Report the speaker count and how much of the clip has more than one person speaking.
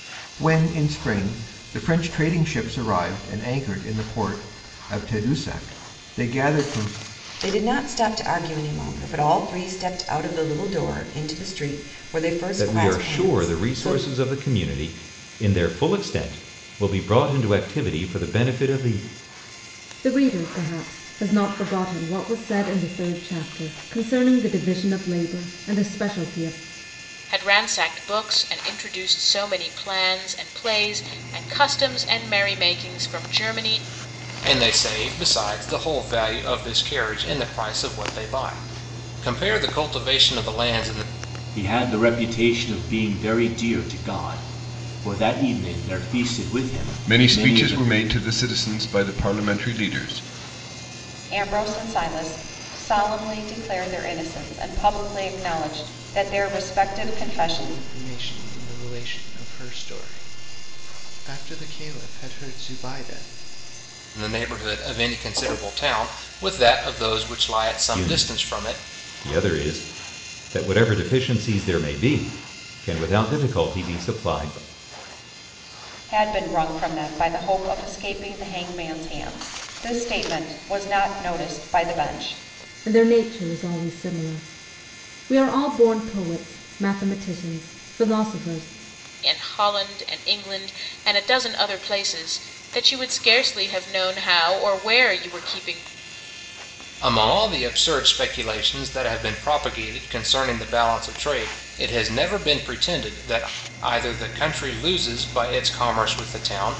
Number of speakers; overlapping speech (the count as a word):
ten, about 4%